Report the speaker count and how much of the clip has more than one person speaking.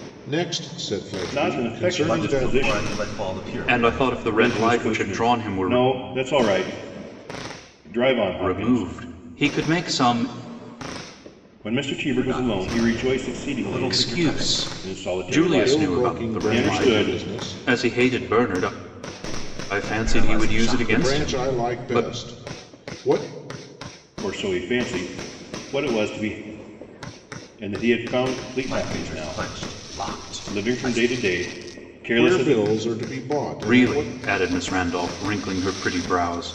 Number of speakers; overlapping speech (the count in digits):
4, about 39%